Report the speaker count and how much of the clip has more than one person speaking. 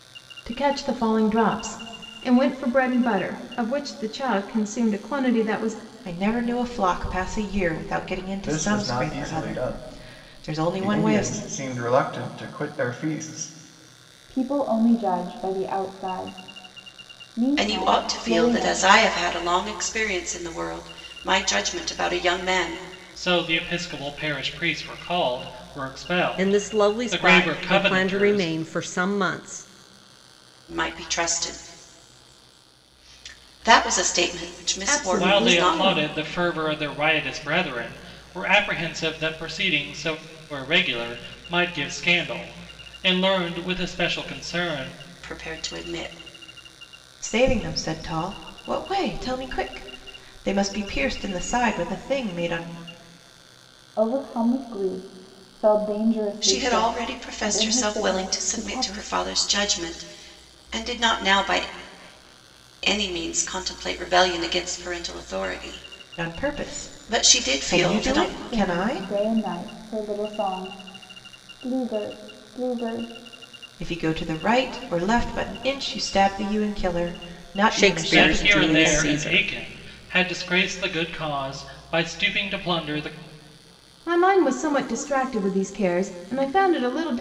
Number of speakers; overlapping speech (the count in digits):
7, about 17%